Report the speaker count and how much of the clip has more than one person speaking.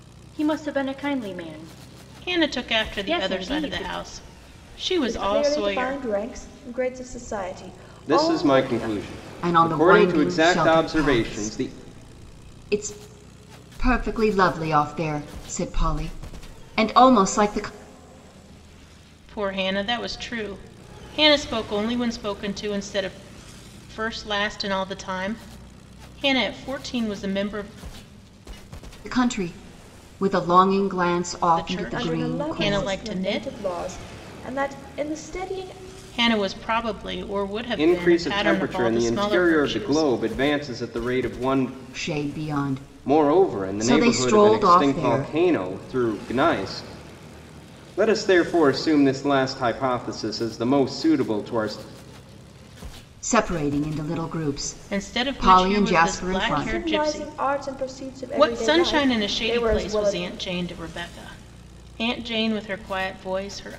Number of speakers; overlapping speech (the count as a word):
five, about 27%